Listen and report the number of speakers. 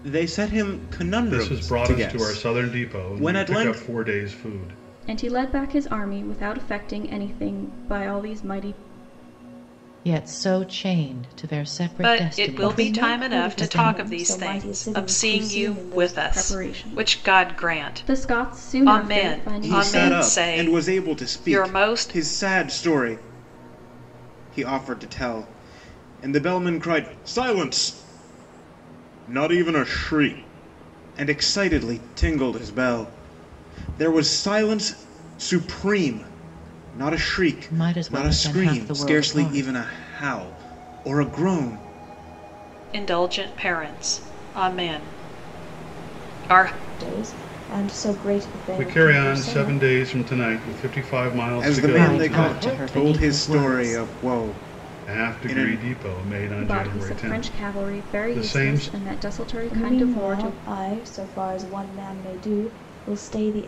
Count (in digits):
6